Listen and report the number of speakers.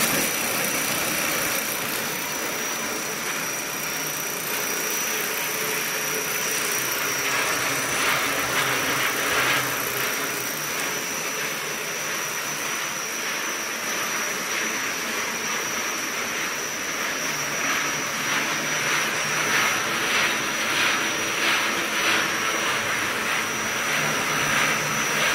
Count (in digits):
0